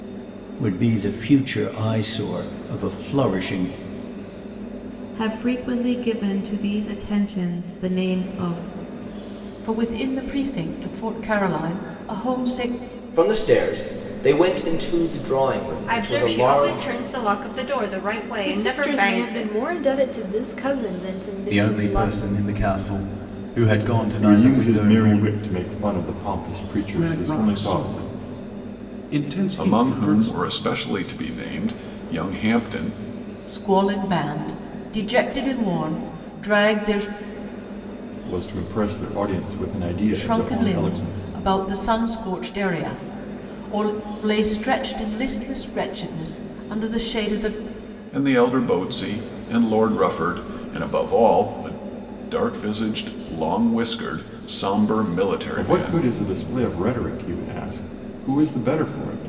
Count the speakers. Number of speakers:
ten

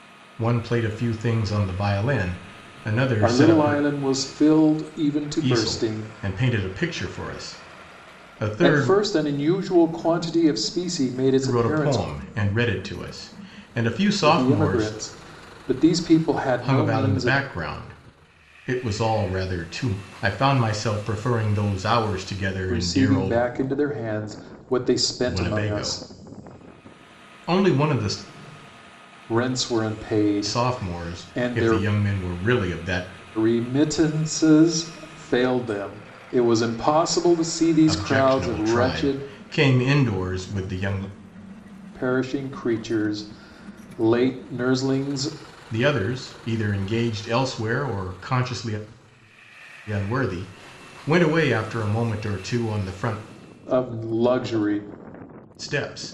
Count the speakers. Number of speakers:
two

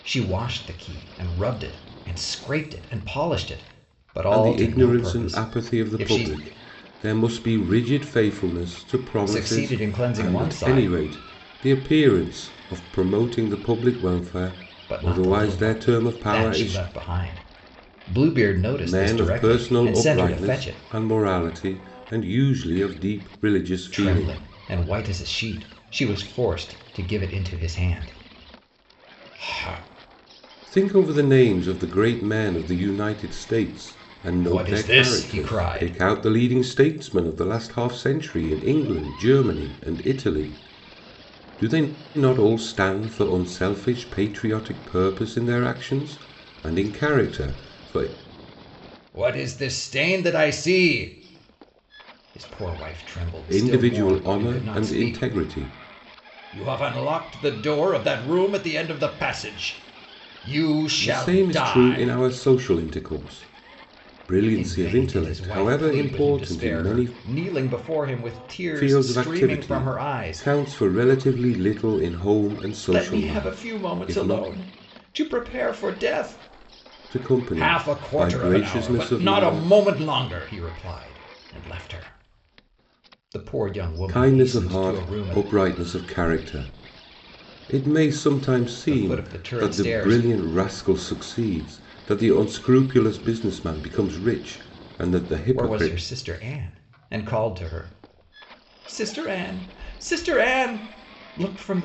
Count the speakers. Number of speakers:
two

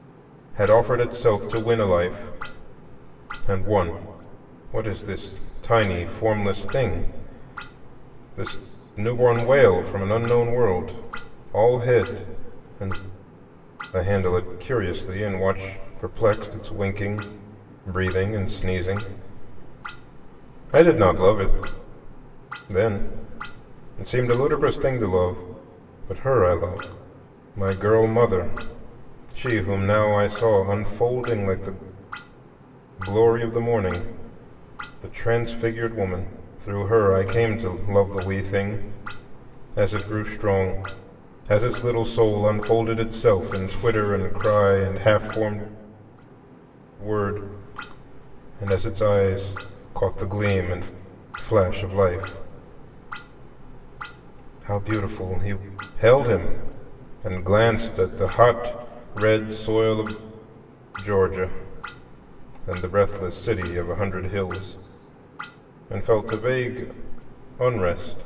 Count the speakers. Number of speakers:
one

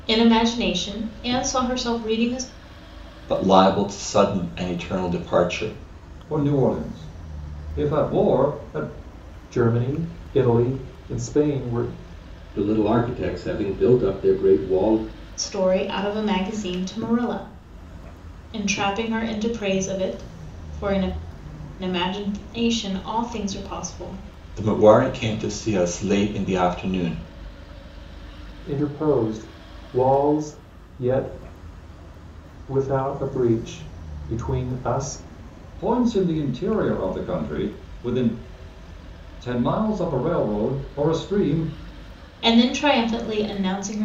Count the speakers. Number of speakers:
five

